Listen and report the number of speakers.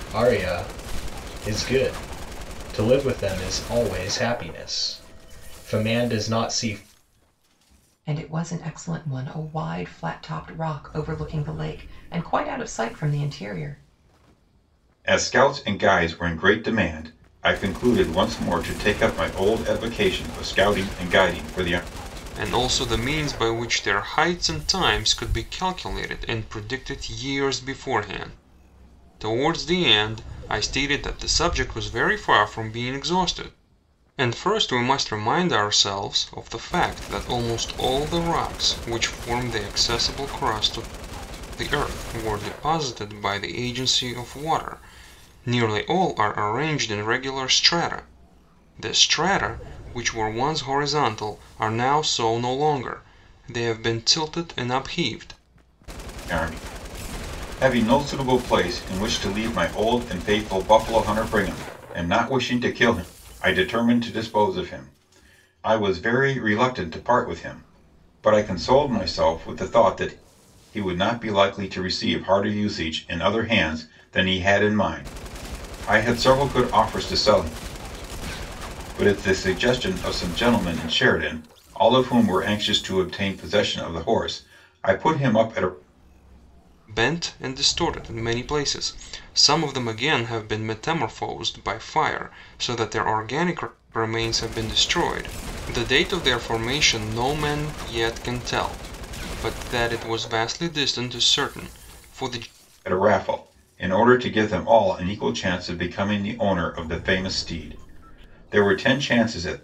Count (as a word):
four